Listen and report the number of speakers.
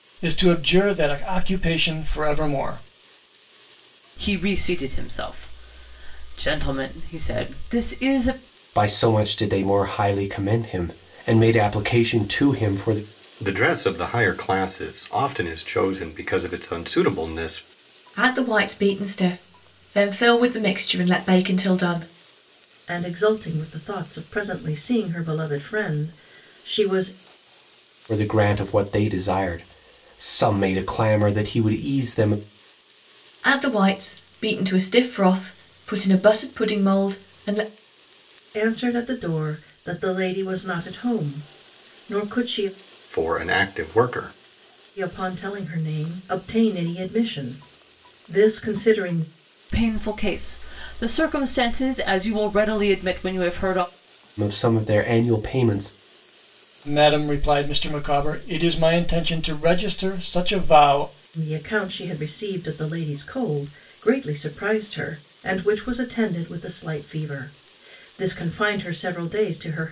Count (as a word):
six